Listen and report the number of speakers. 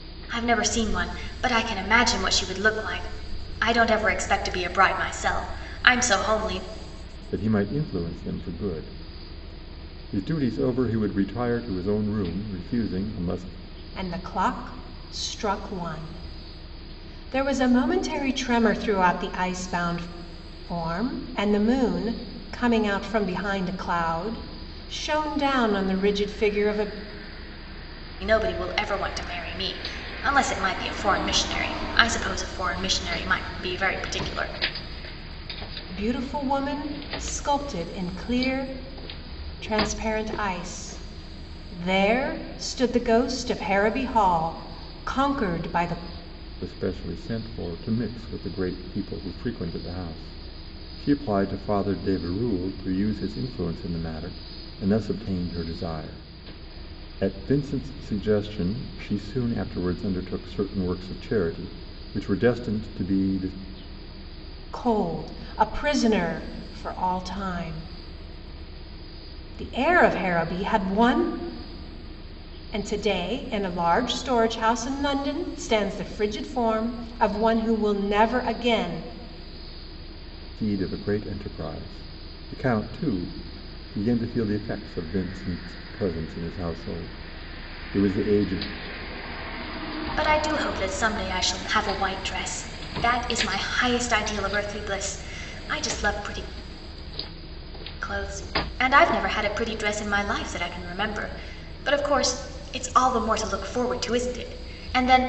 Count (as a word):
three